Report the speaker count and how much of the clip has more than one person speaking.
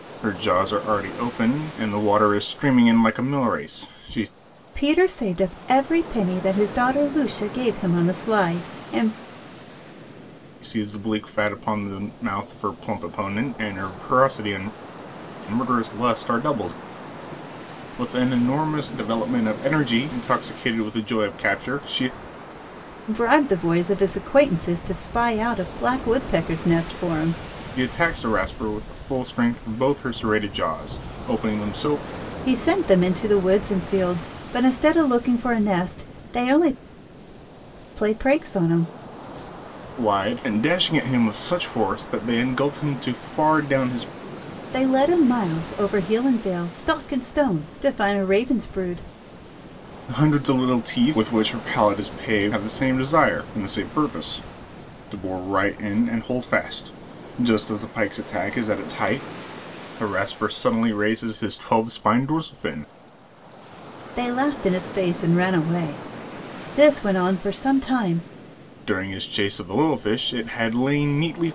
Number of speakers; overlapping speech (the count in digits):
2, no overlap